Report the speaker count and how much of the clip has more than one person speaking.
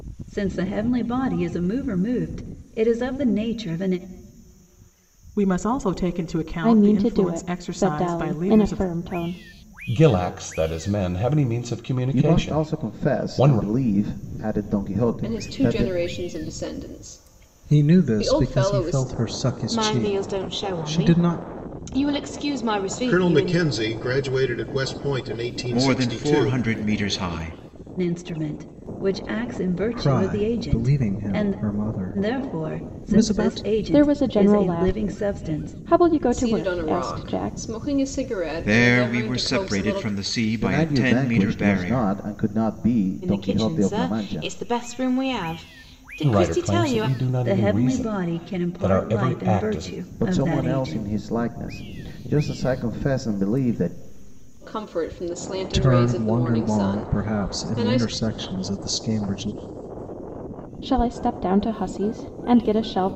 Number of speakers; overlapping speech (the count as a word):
ten, about 43%